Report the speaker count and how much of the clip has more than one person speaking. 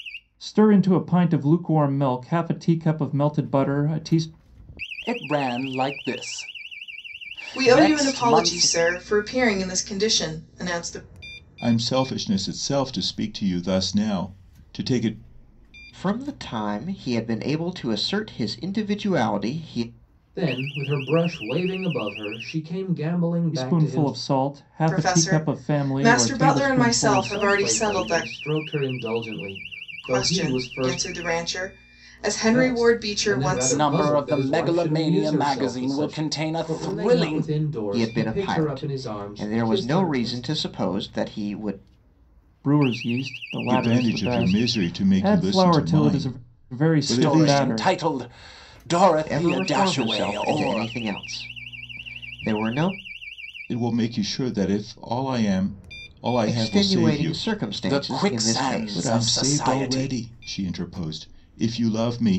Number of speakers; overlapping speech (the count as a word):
six, about 36%